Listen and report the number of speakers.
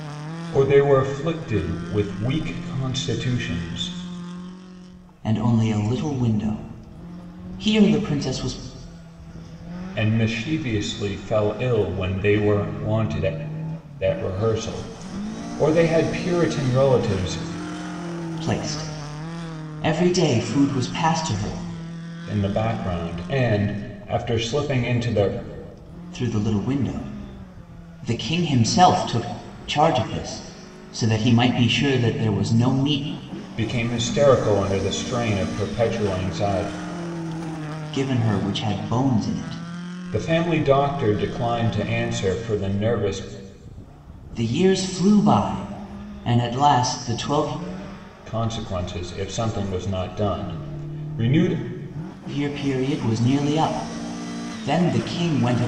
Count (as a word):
two